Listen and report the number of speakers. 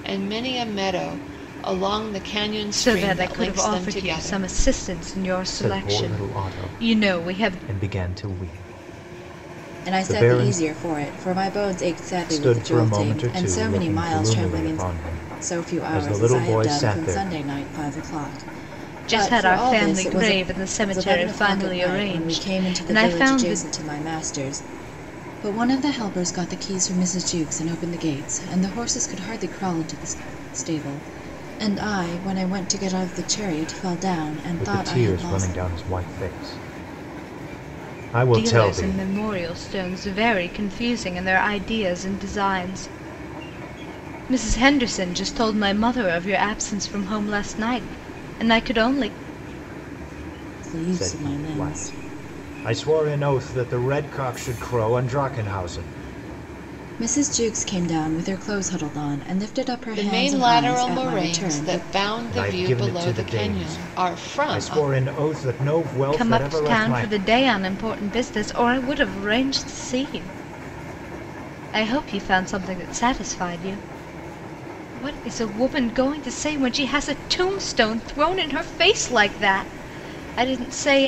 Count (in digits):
4